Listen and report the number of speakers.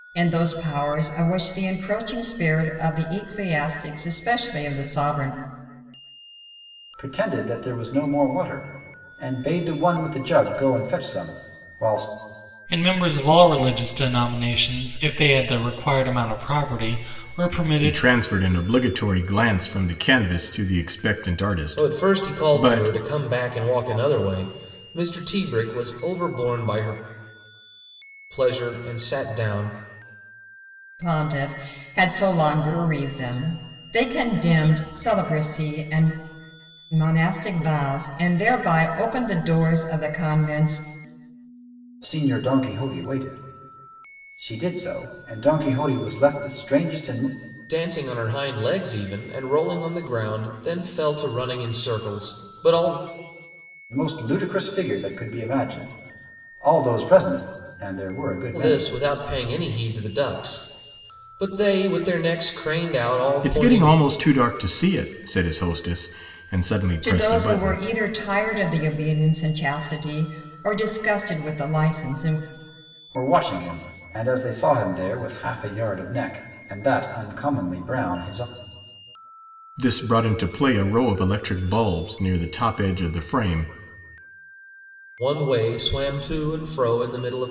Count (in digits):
5